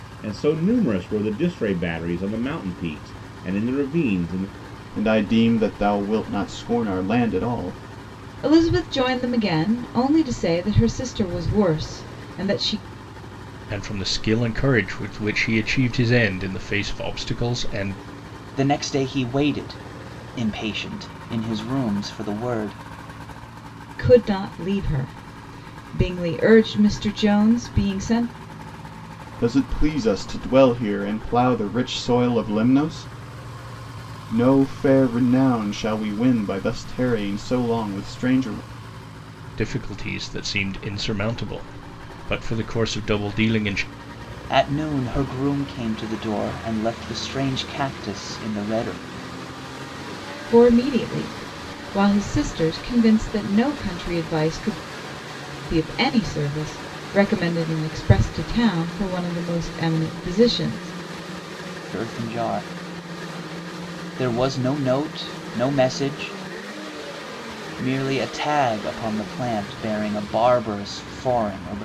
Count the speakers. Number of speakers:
five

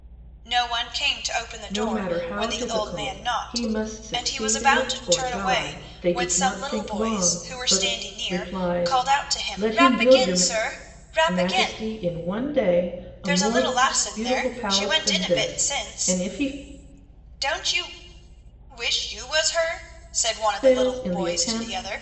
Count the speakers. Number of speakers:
two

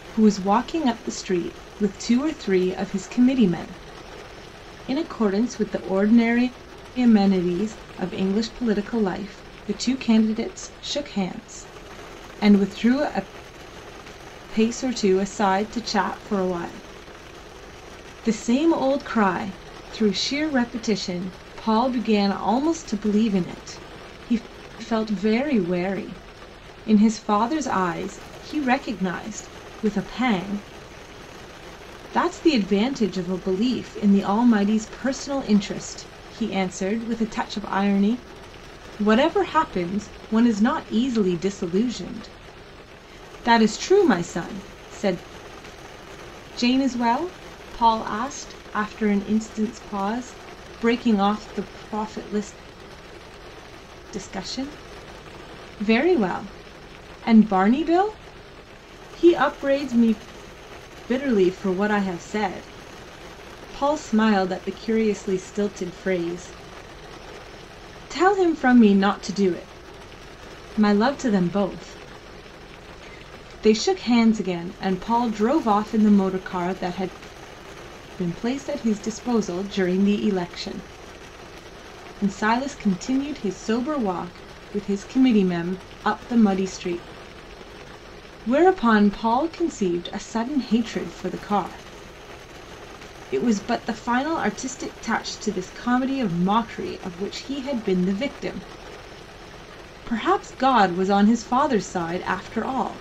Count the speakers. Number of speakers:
one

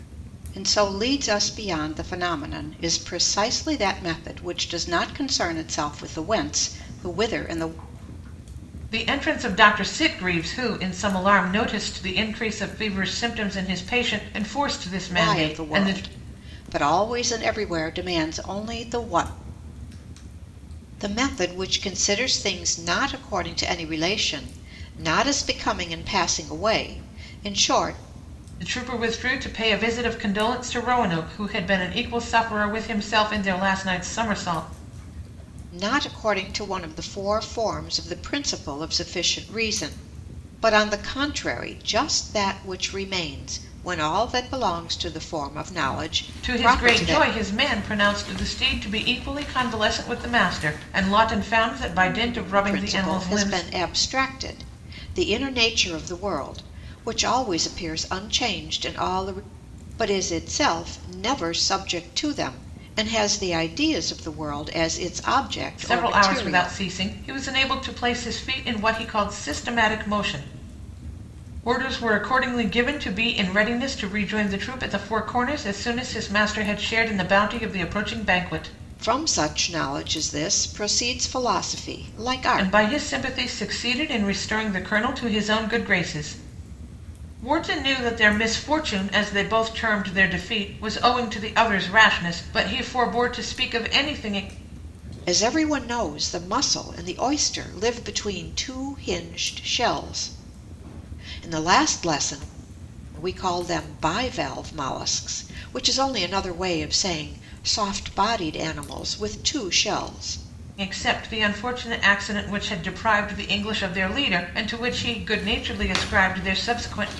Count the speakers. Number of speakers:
two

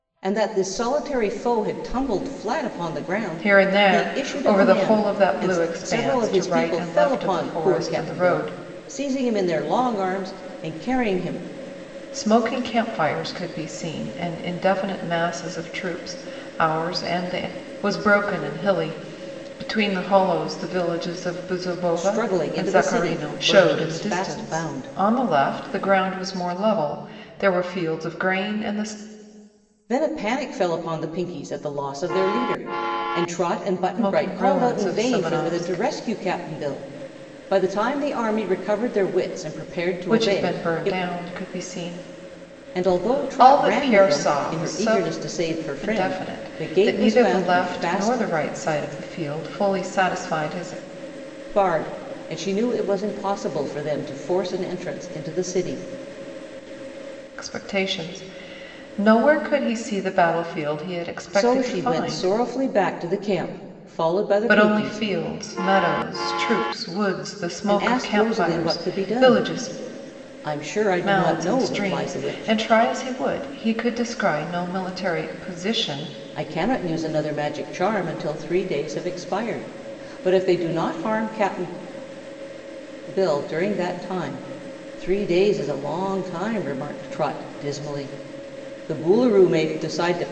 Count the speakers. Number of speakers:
two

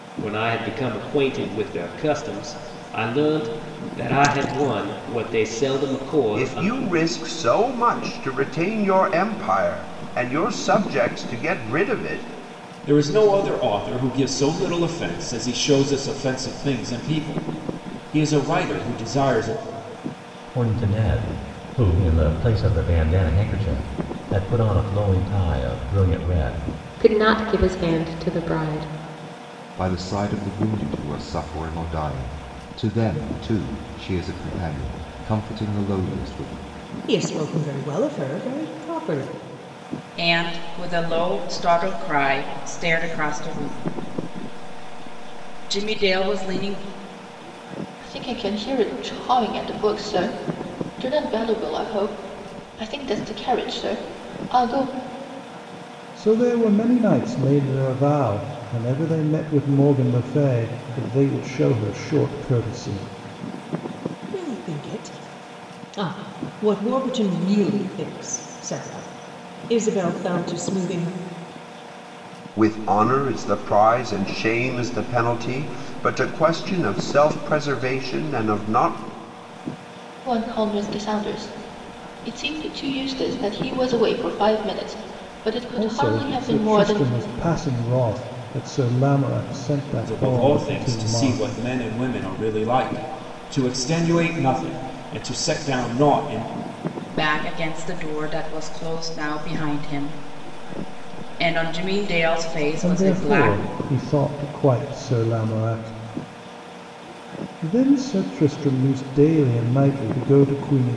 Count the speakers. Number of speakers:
ten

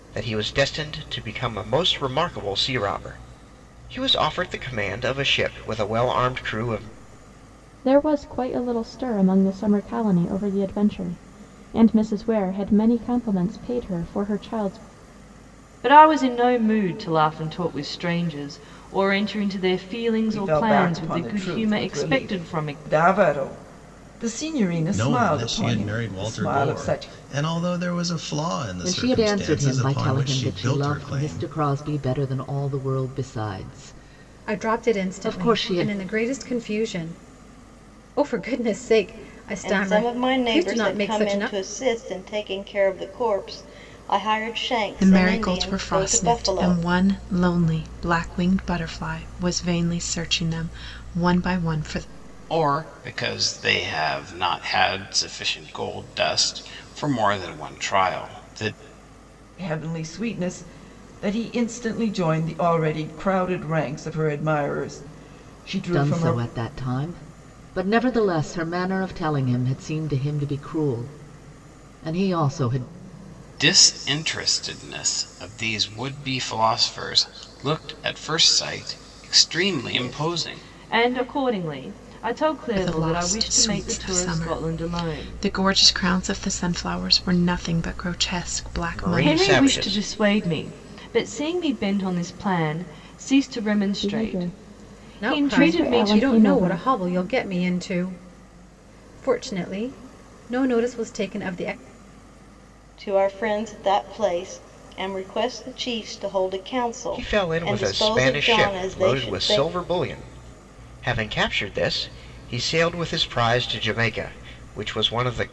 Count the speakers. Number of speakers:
ten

